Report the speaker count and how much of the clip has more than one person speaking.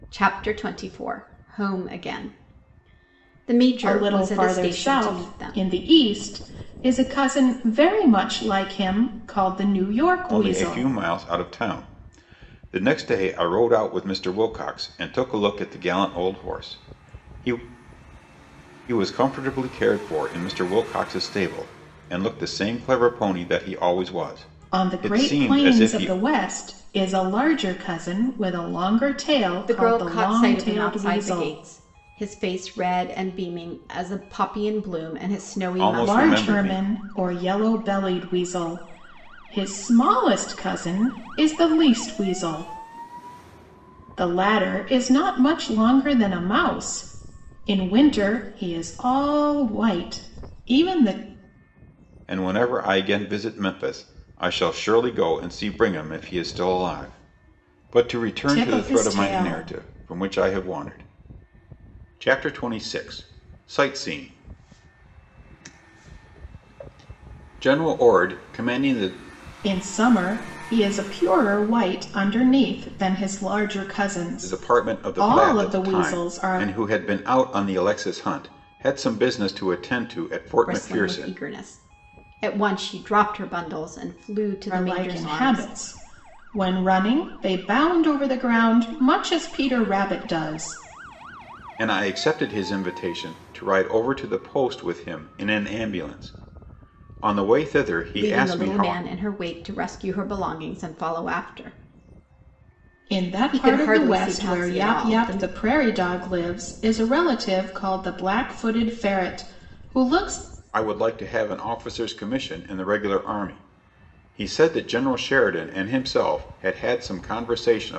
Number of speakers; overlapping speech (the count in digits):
3, about 13%